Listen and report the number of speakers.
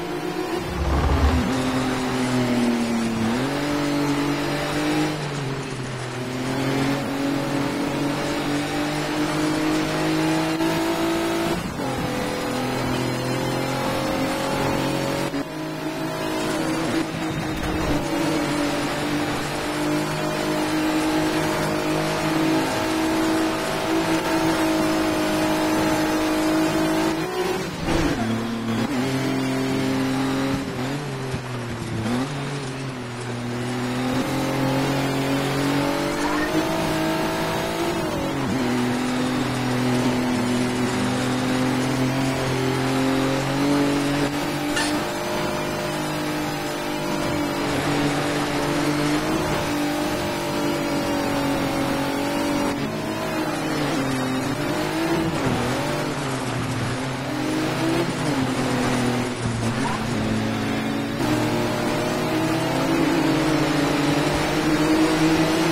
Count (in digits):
0